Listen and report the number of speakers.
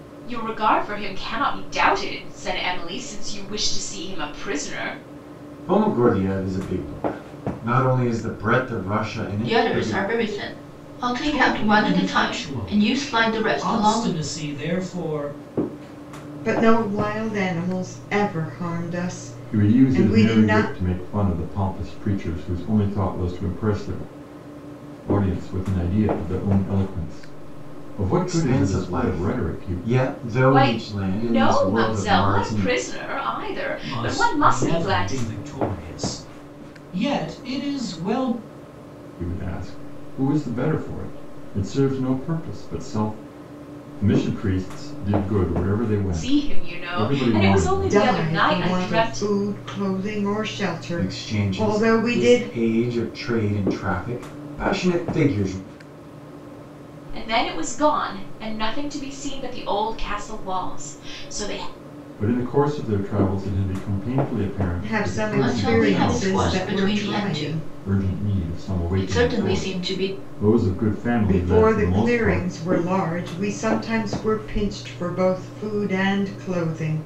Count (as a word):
six